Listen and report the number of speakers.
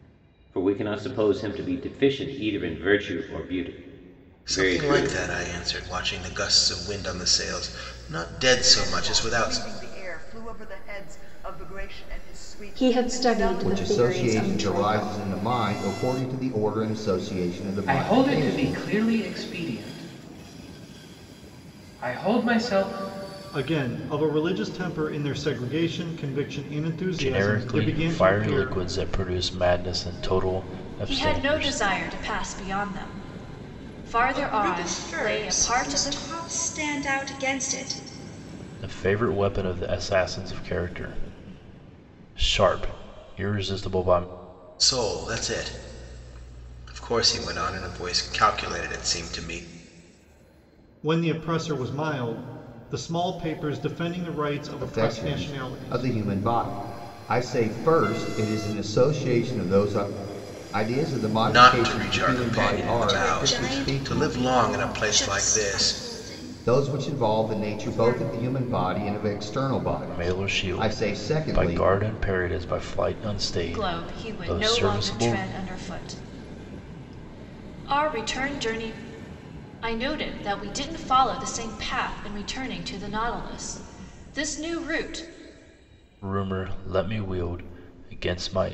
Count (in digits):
10